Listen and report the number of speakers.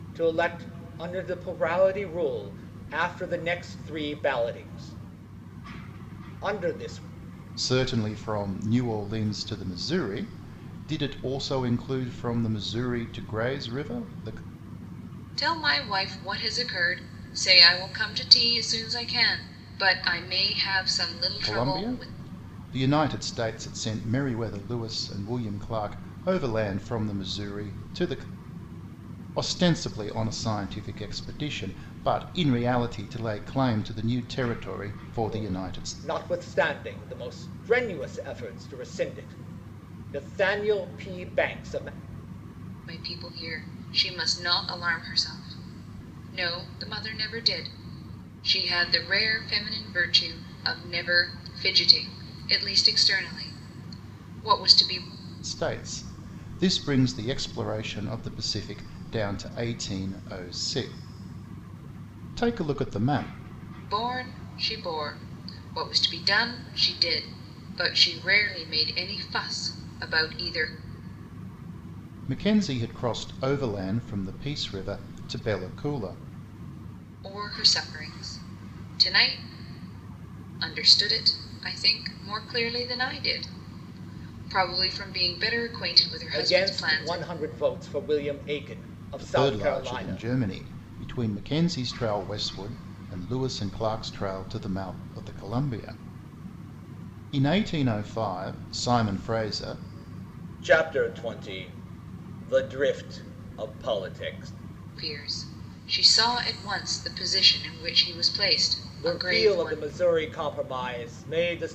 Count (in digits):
3